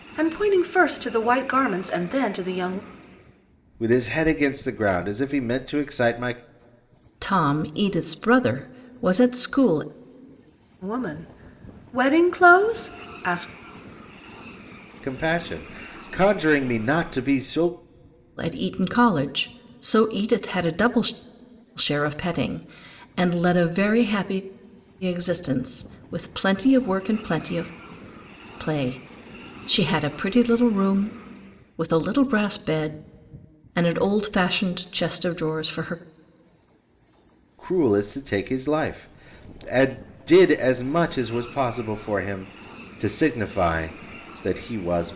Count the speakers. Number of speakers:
3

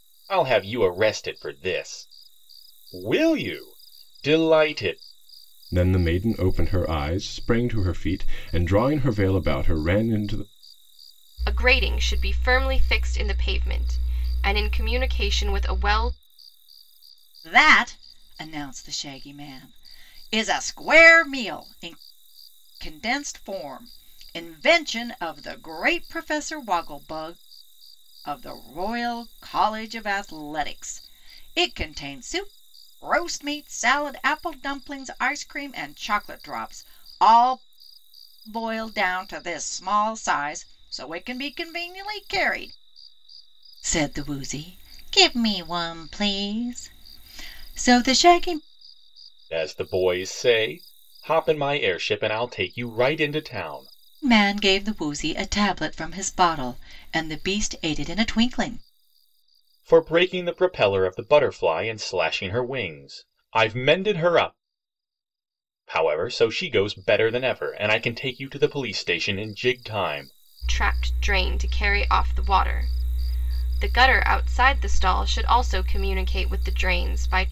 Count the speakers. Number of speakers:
4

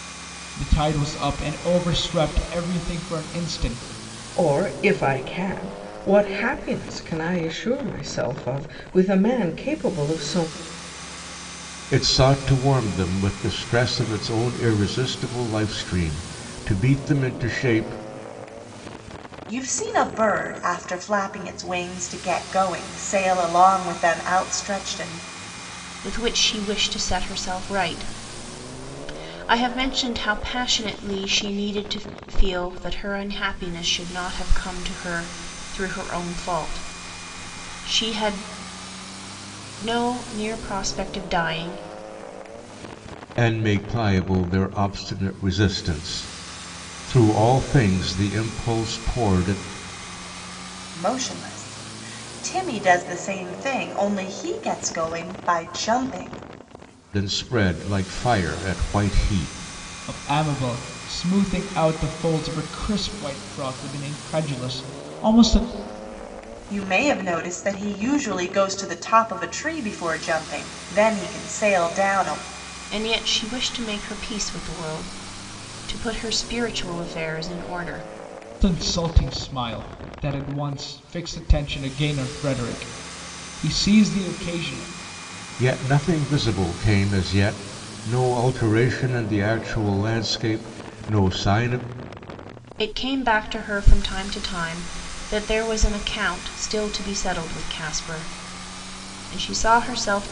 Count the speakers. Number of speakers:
5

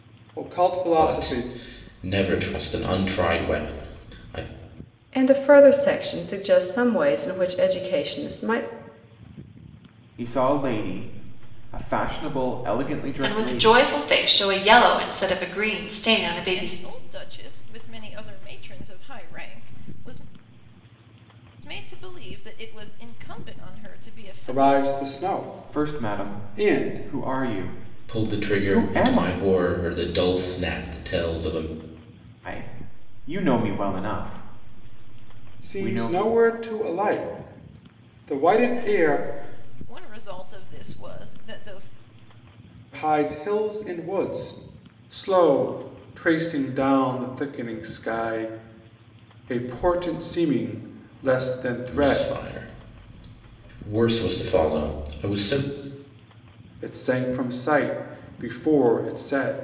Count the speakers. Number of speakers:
6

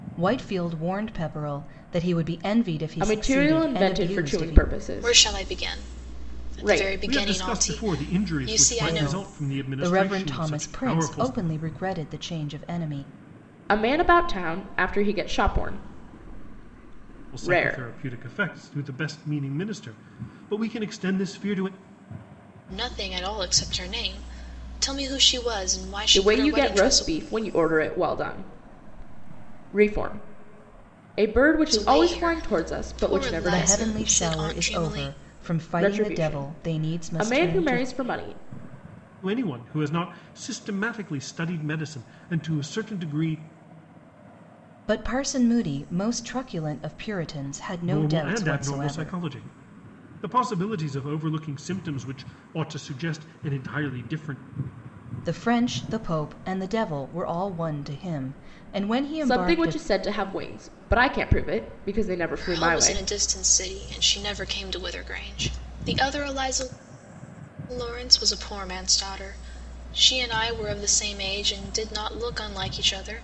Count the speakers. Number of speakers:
4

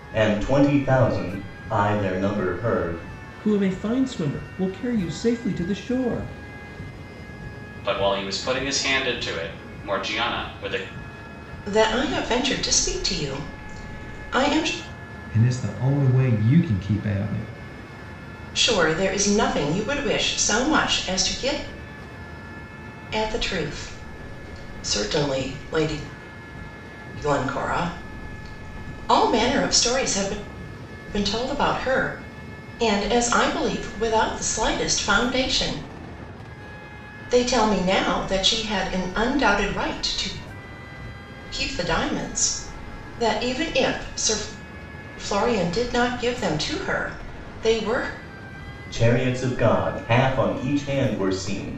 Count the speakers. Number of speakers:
5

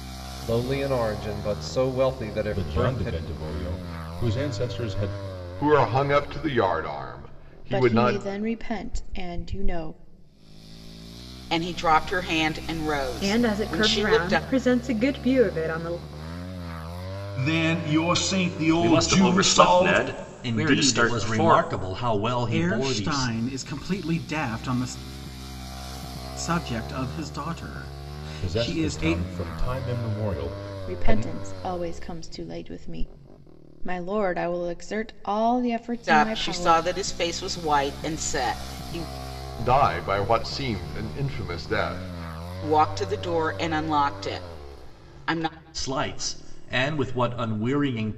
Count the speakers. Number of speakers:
10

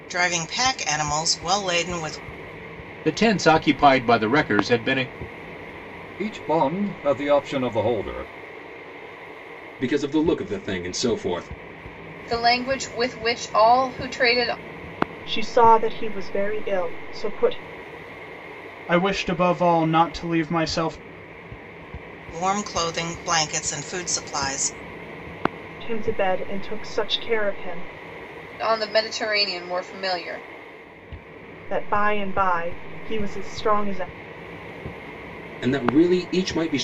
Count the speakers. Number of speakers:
7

